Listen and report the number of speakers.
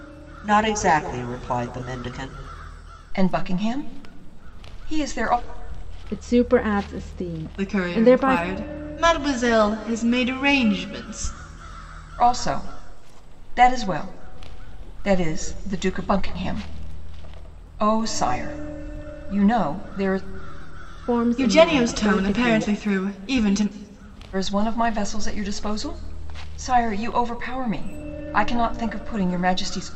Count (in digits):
4